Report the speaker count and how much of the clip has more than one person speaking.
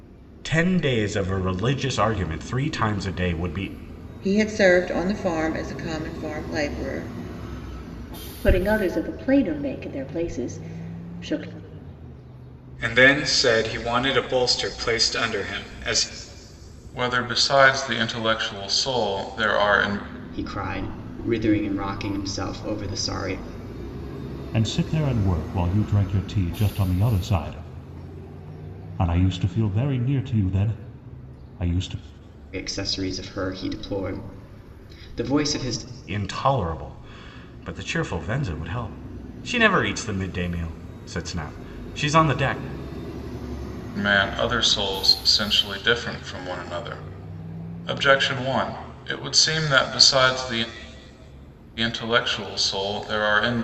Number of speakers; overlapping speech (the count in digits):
7, no overlap